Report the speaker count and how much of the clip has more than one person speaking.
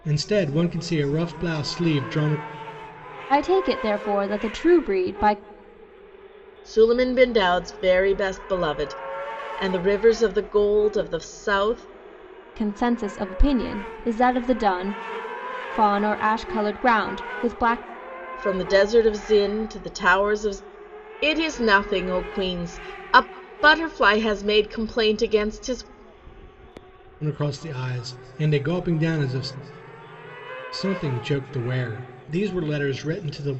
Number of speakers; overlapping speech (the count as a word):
three, no overlap